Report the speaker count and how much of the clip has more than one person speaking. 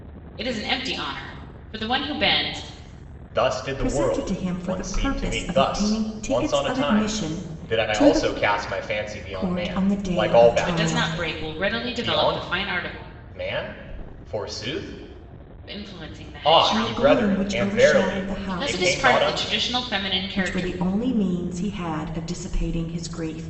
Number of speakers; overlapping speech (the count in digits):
3, about 48%